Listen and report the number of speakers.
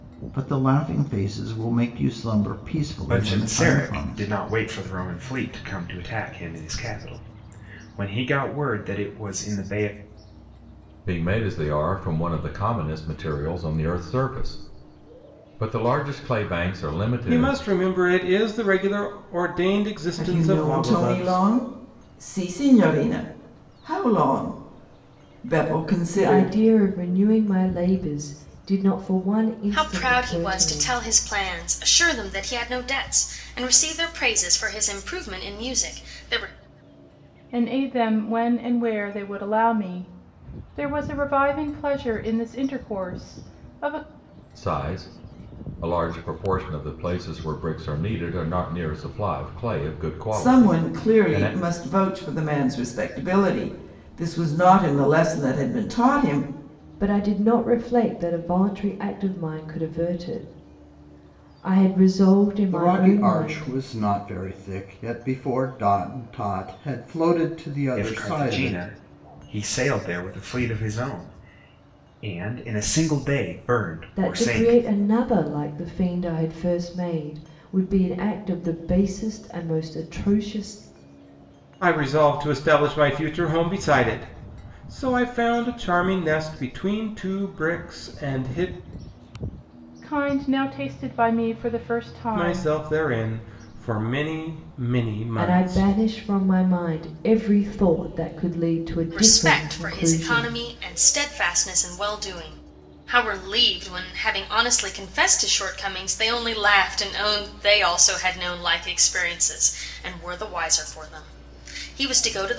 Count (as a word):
eight